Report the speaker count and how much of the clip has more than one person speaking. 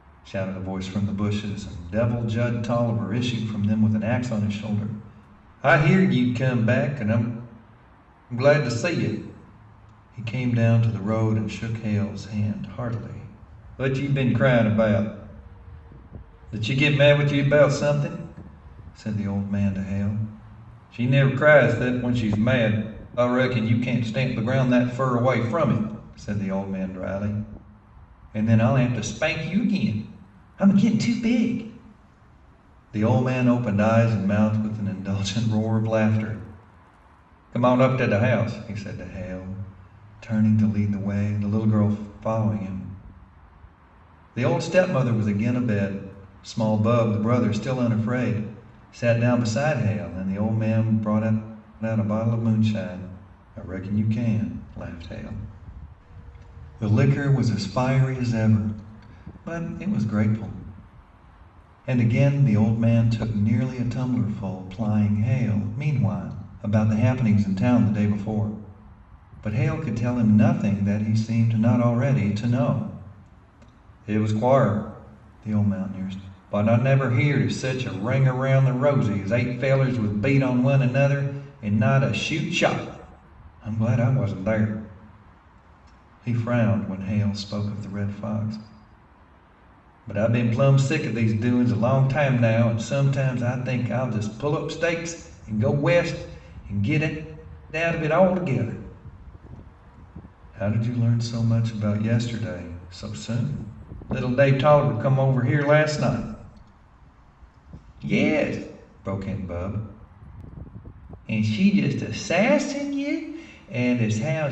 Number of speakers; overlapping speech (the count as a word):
one, no overlap